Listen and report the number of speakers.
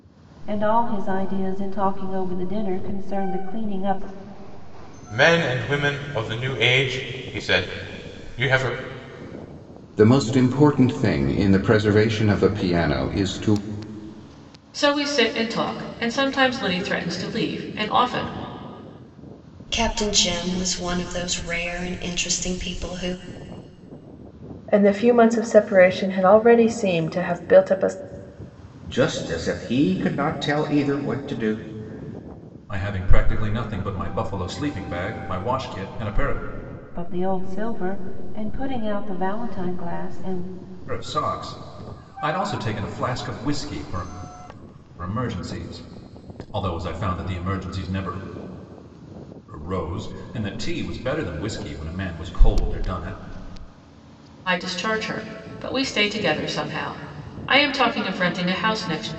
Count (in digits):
8